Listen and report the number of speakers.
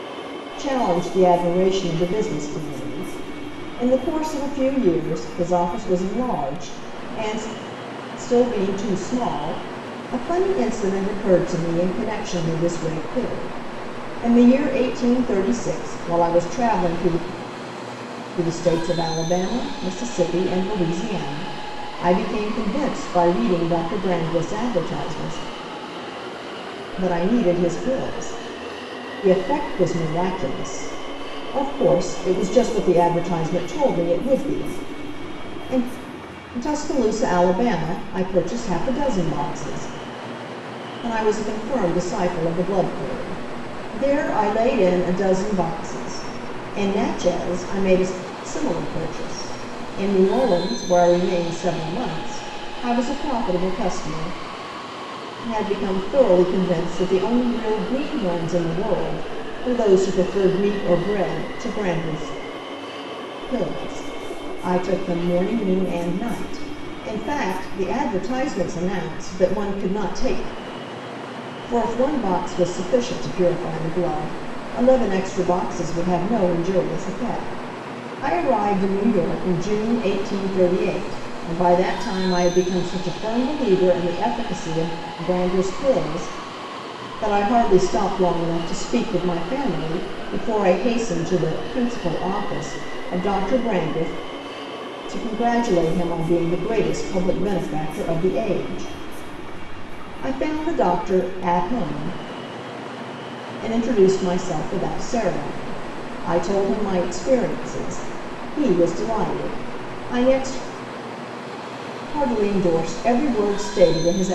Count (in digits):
1